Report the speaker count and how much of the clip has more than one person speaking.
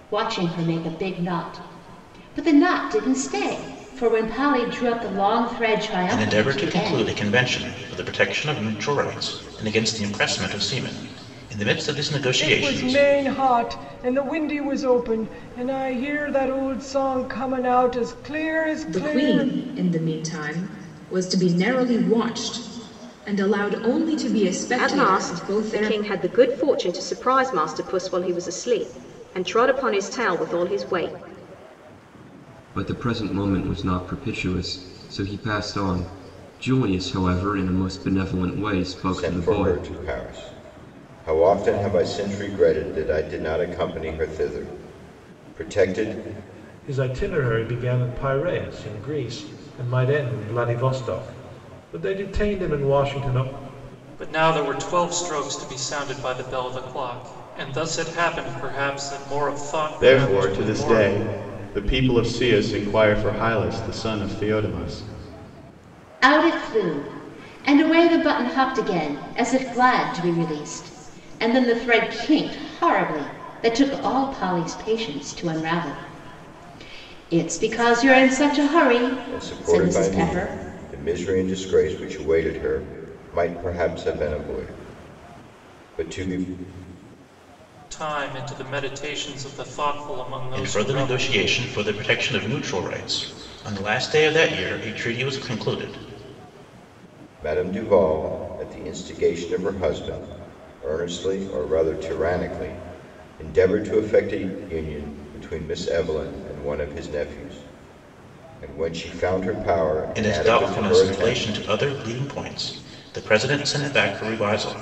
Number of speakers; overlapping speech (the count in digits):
10, about 8%